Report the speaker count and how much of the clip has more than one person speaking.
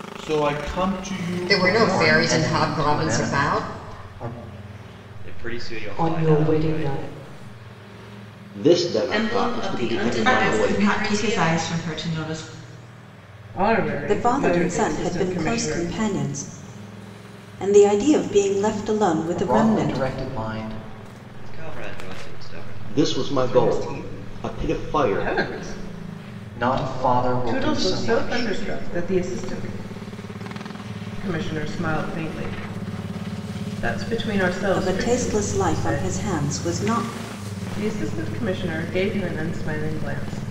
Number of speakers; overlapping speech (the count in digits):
10, about 36%